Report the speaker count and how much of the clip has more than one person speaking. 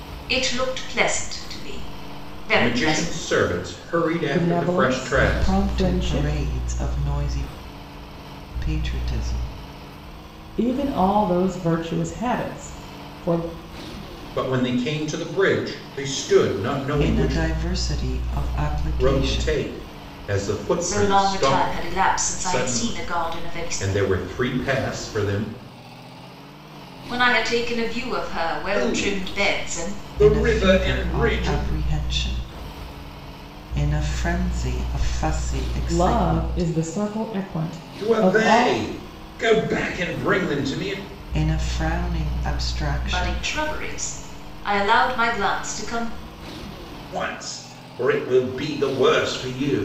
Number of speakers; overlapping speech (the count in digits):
4, about 22%